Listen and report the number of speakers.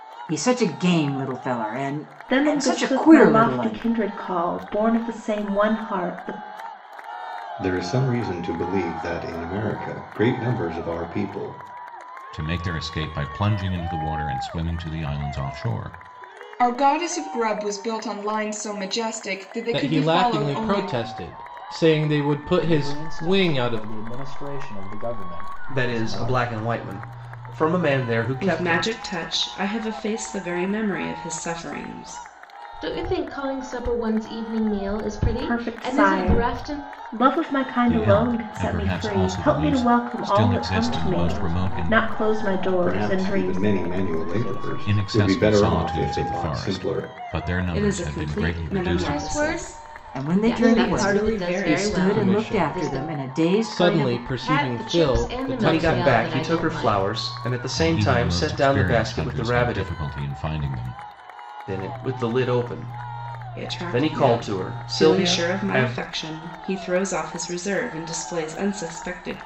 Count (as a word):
ten